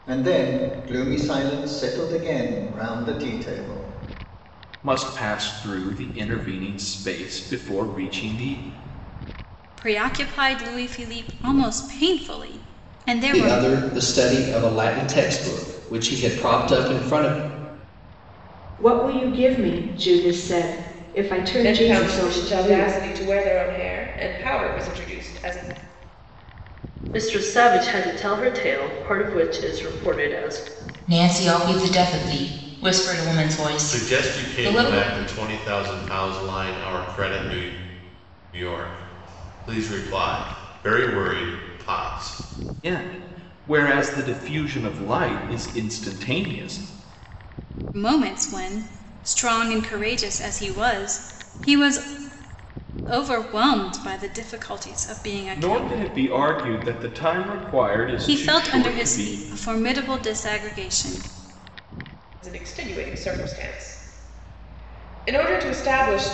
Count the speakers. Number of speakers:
nine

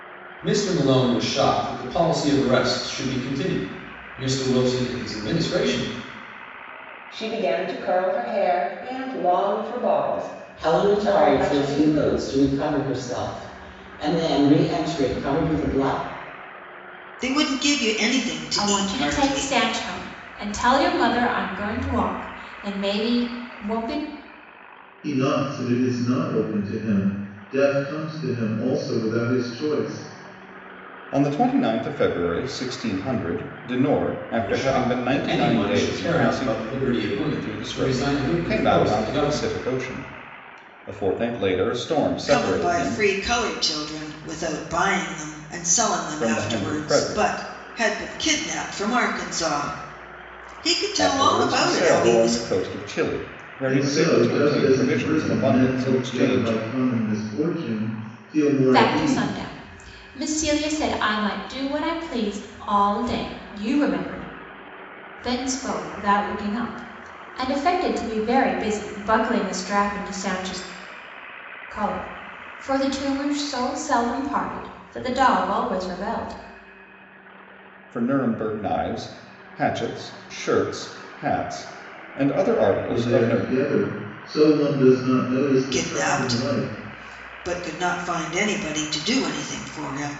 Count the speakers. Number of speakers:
seven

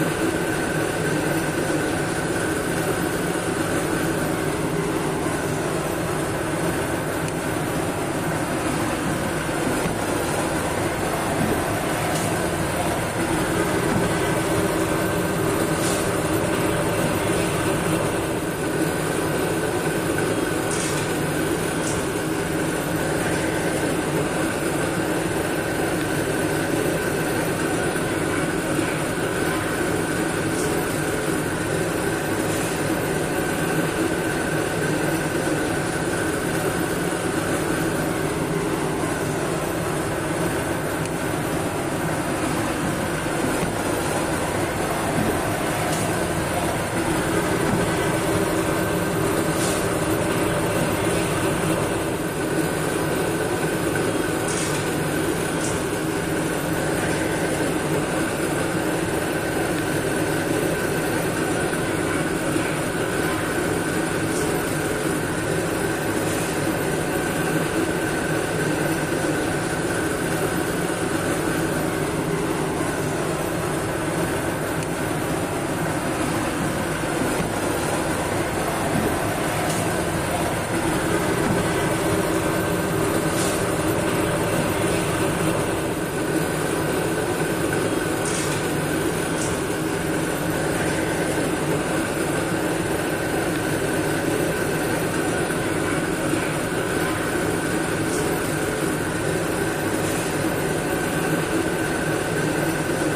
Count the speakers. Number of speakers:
zero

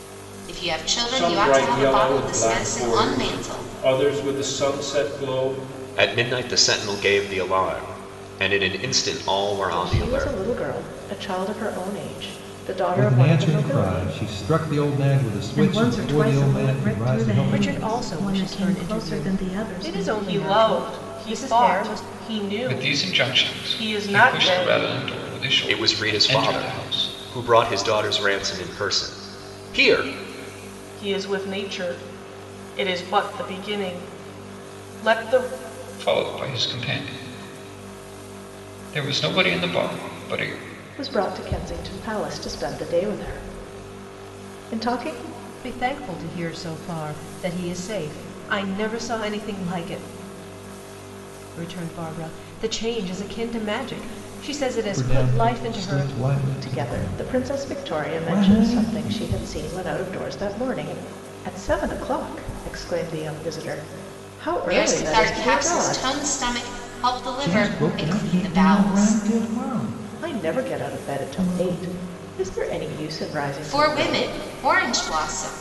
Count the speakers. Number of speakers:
nine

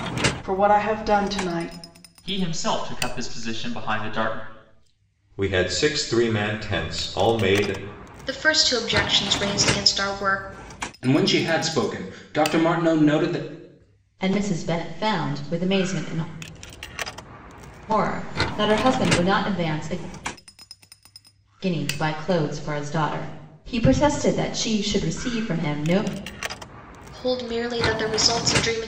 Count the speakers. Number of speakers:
six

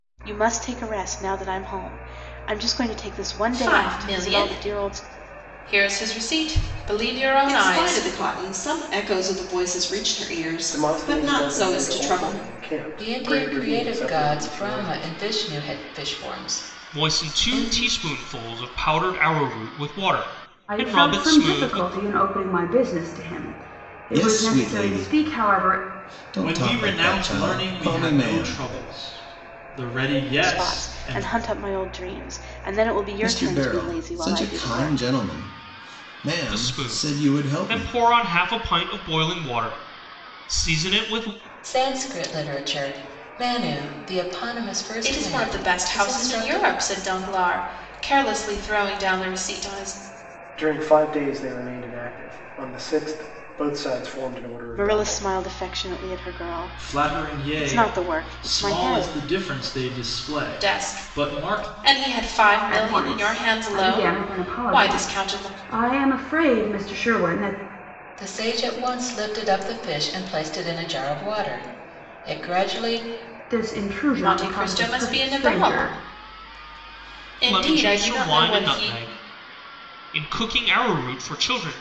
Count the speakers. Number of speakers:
nine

